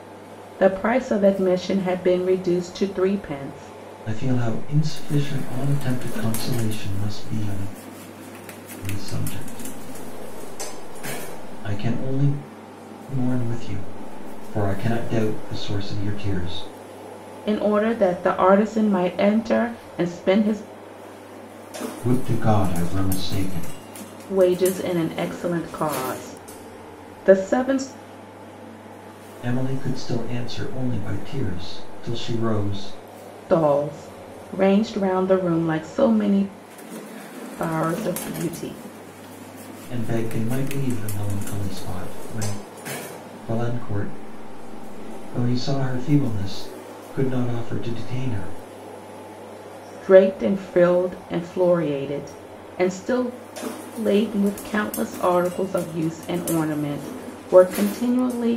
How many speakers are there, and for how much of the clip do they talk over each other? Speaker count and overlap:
two, no overlap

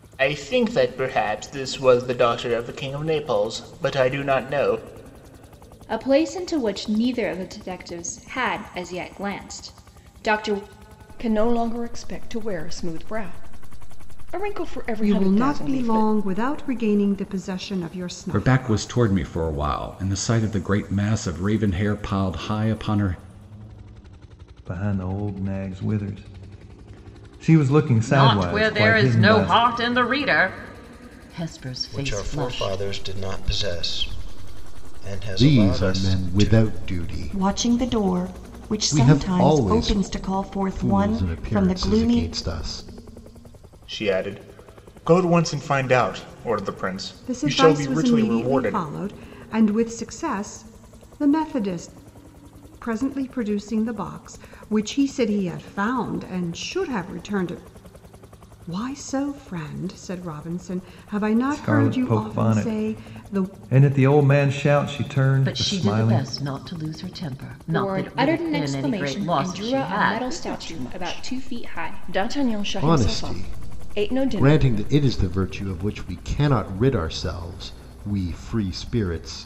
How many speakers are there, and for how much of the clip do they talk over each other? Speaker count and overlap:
ten, about 26%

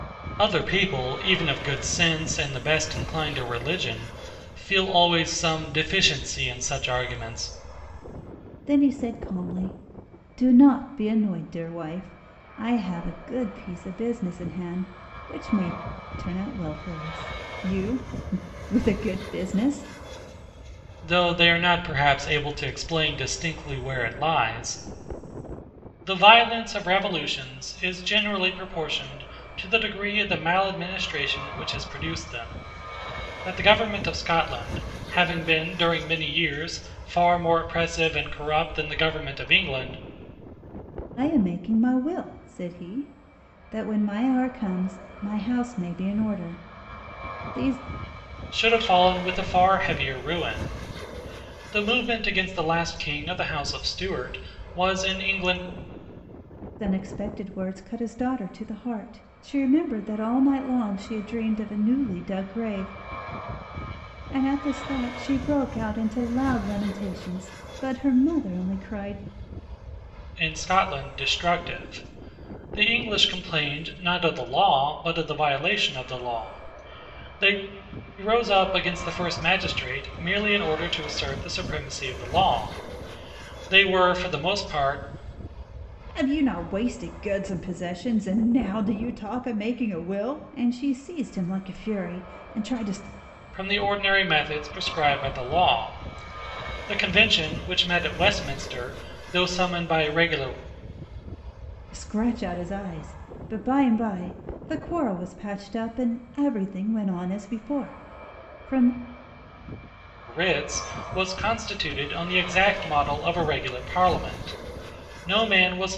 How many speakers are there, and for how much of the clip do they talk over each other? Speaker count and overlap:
two, no overlap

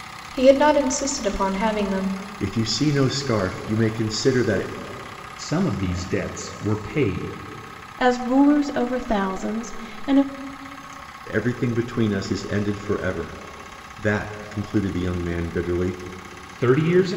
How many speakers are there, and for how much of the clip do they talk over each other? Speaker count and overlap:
four, no overlap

